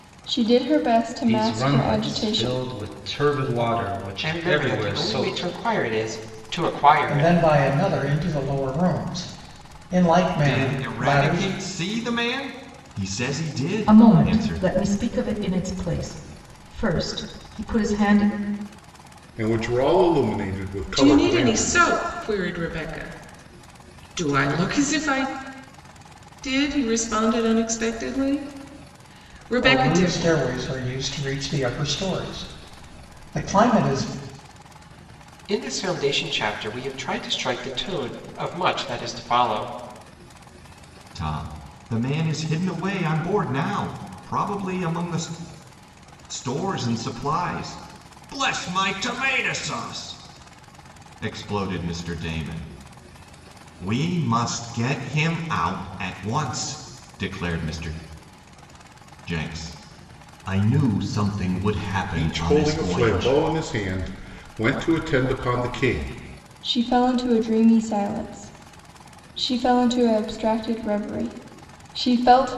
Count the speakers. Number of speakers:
eight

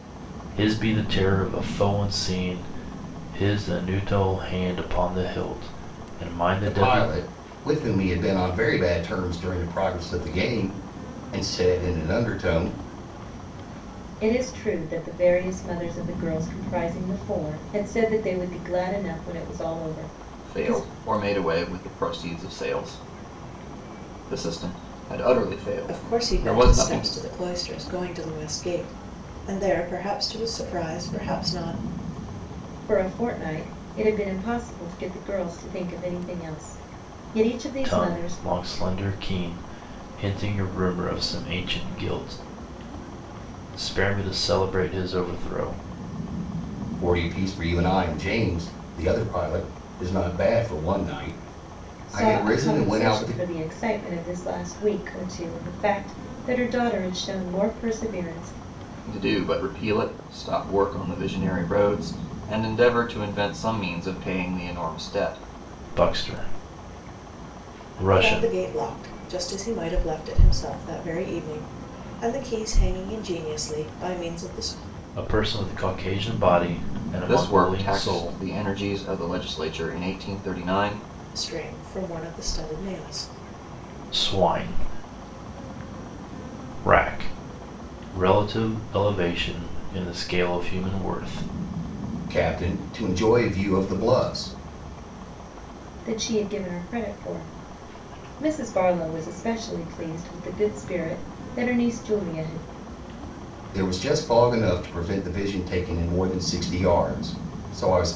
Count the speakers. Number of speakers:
five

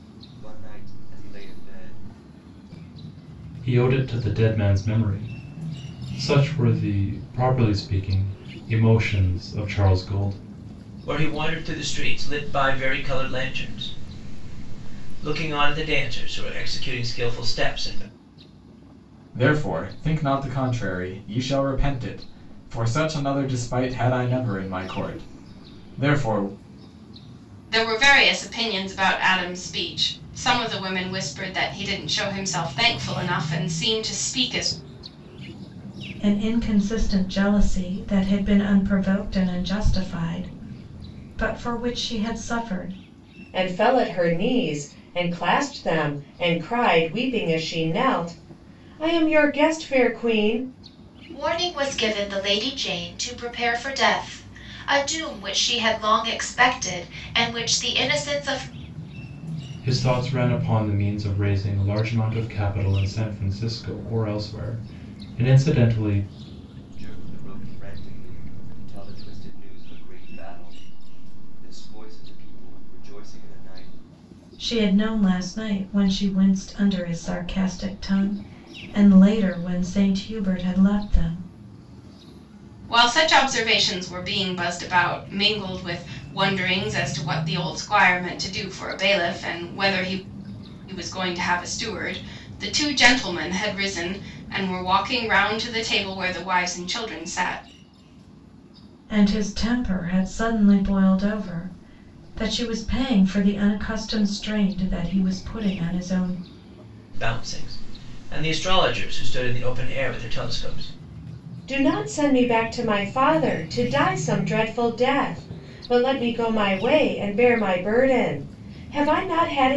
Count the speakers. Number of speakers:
eight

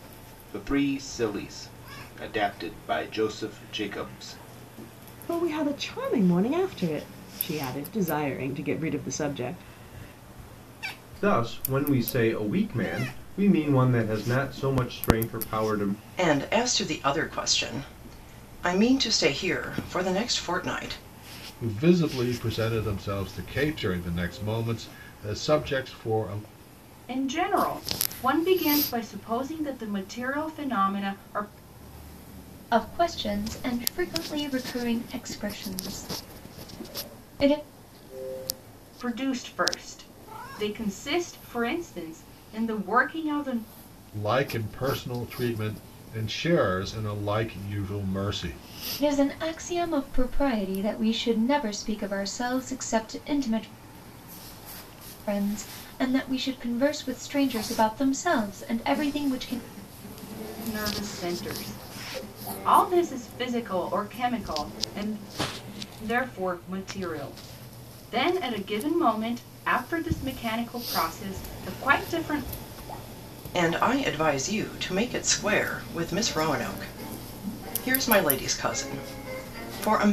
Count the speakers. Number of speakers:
seven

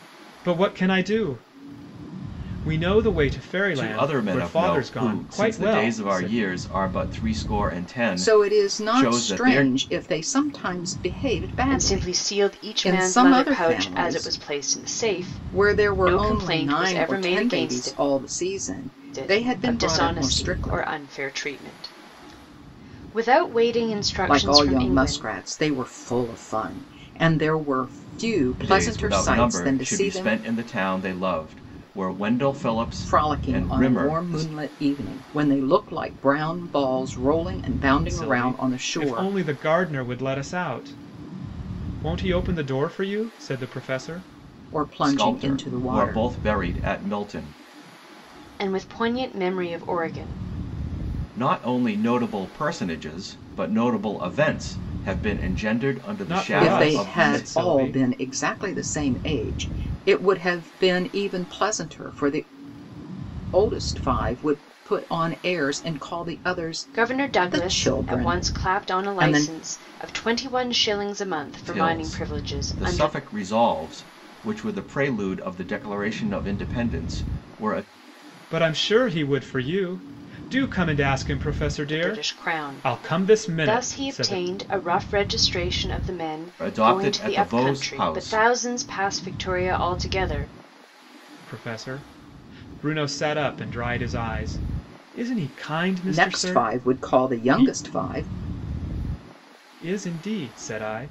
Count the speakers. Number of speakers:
four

